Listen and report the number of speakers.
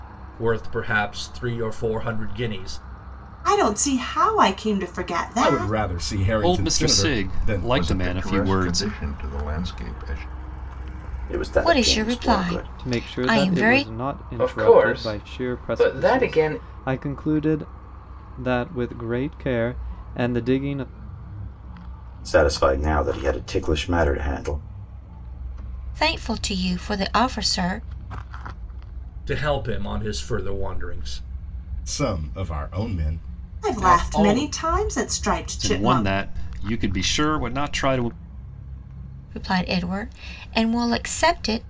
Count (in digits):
9